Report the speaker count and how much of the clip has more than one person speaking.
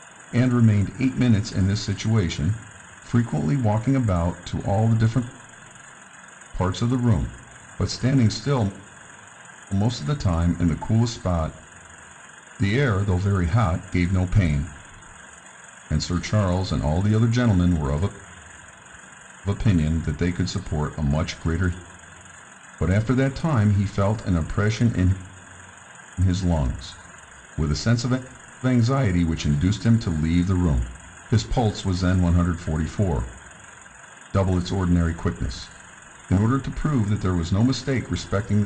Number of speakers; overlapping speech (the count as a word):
one, no overlap